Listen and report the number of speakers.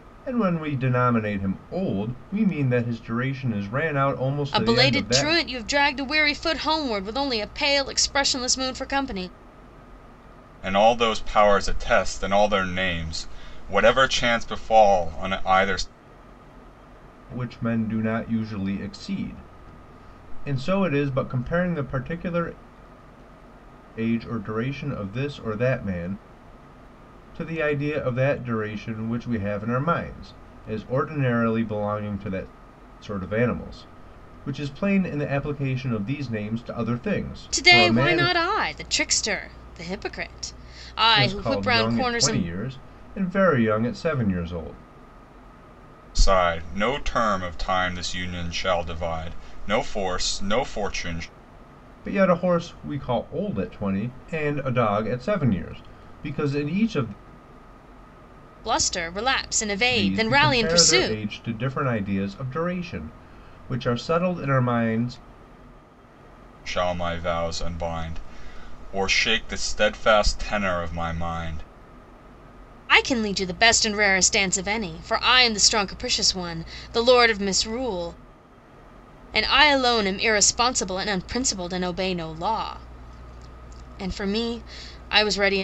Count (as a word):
three